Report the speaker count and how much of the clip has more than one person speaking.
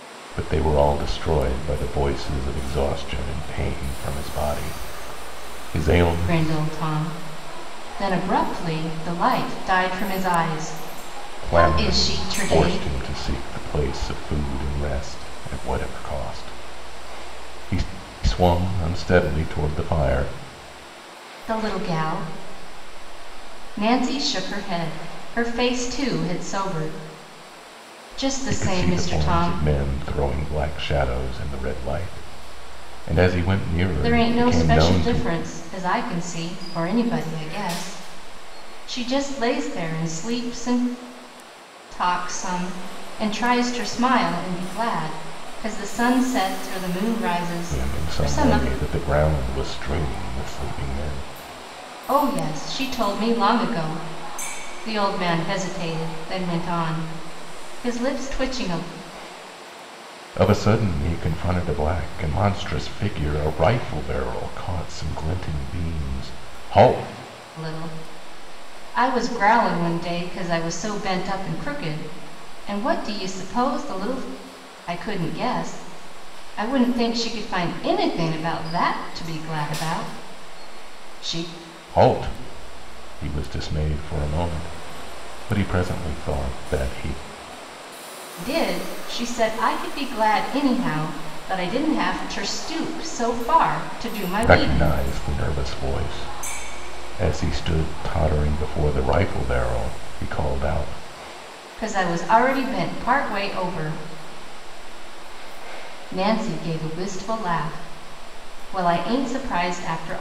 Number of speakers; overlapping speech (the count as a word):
two, about 5%